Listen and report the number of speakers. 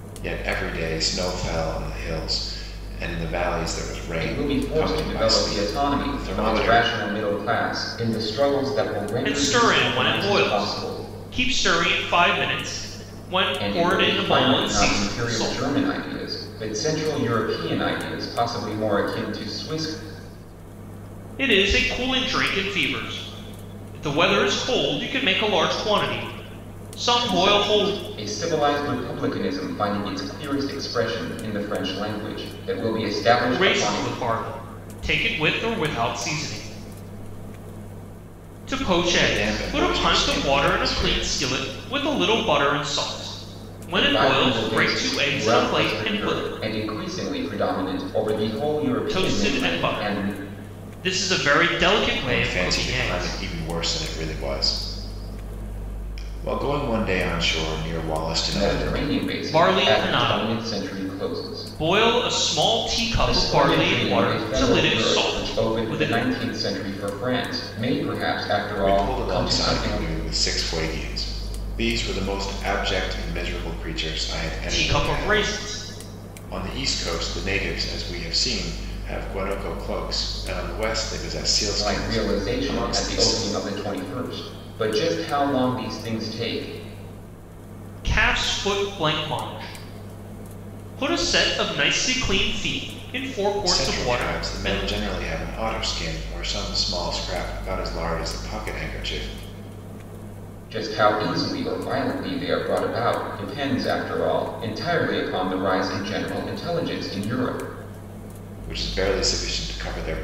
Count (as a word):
three